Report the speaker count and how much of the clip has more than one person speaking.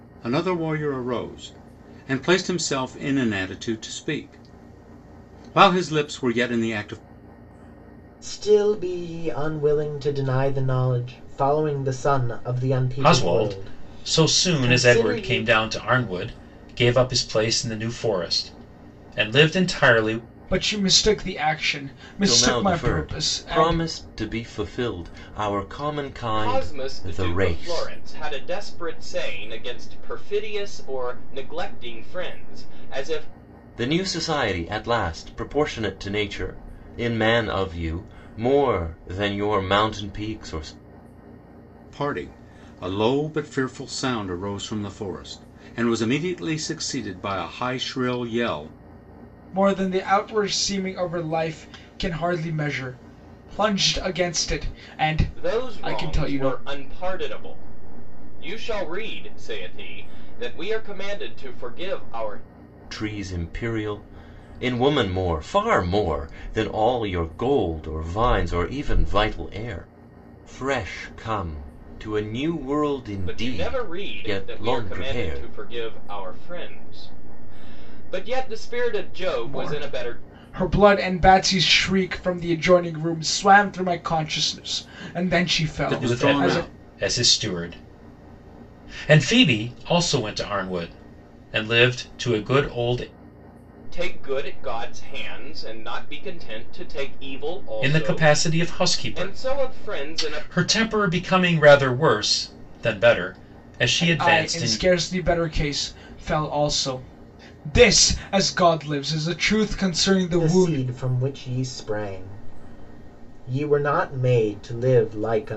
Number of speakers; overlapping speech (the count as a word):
six, about 13%